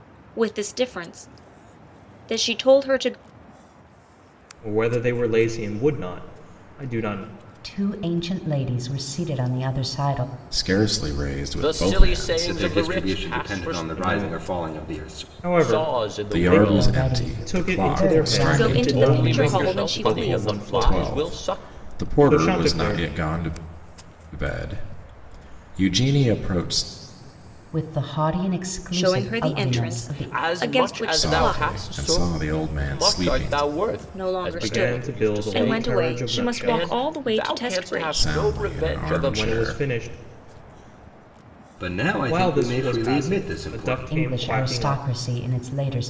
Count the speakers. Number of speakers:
6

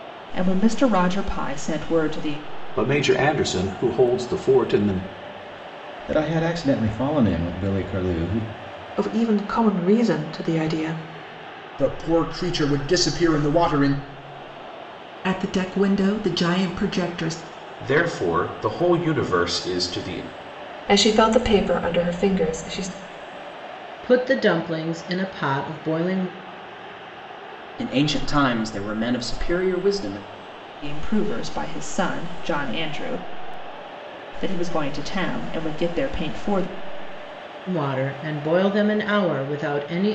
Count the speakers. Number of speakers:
10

